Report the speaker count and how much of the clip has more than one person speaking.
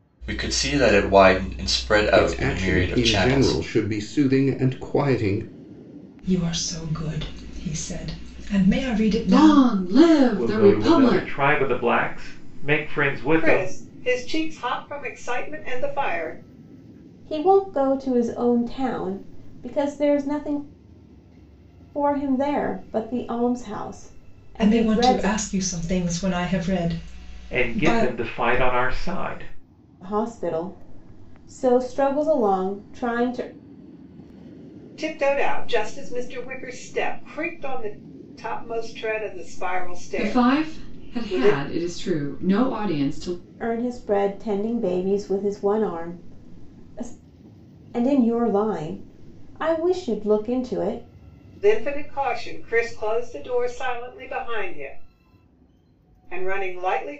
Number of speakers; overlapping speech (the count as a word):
seven, about 11%